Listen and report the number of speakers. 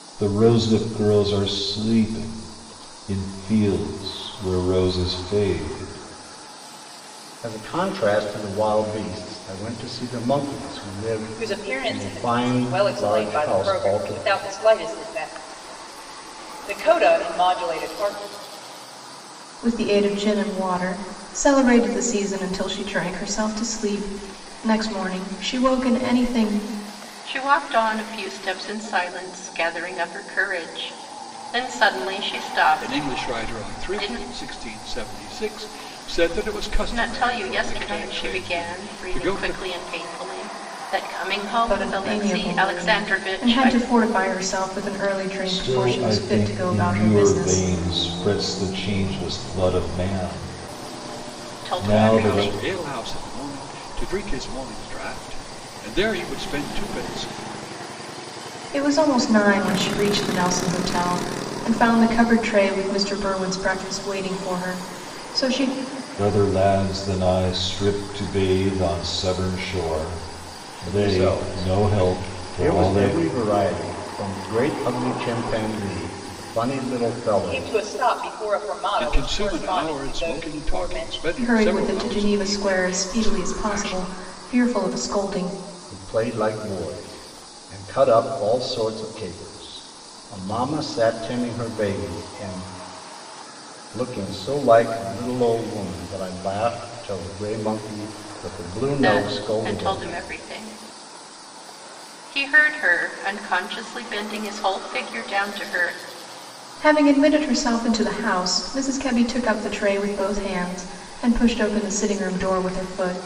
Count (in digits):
6